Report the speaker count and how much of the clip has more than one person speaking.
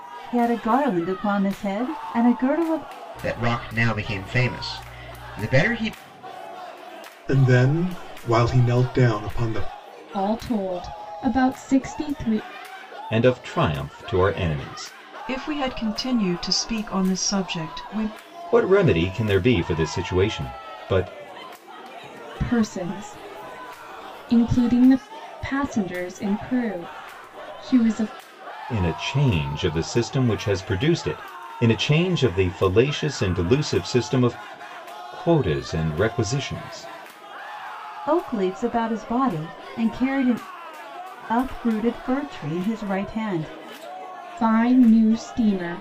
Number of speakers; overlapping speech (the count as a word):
six, no overlap